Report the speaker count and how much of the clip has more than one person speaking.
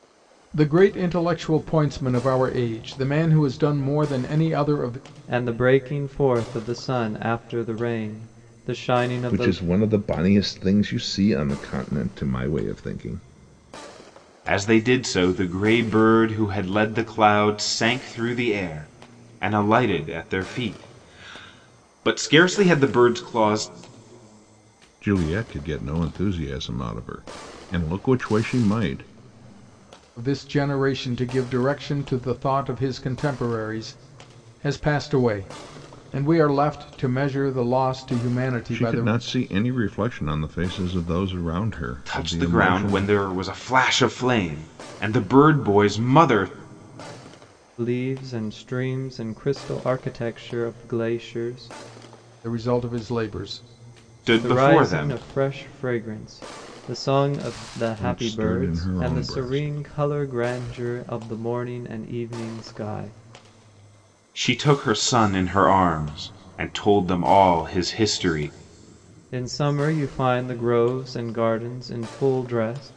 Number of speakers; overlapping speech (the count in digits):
4, about 6%